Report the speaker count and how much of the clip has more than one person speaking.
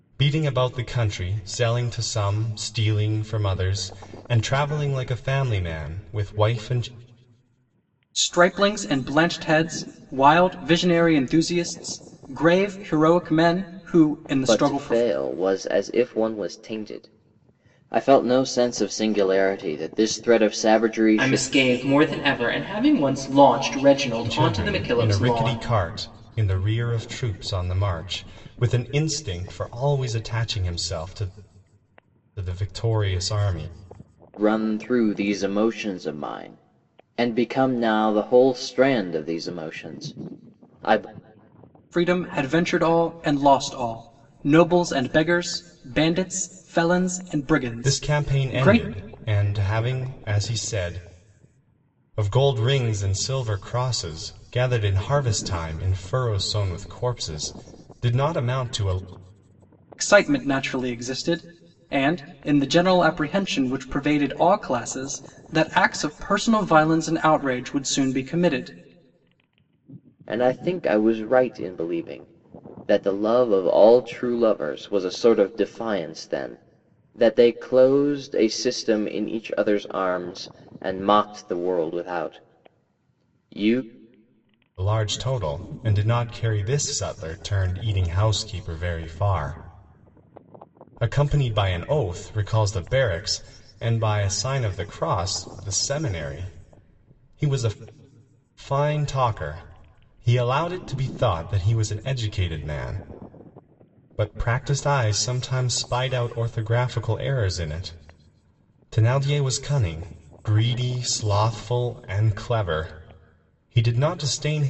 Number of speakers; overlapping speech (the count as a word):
four, about 3%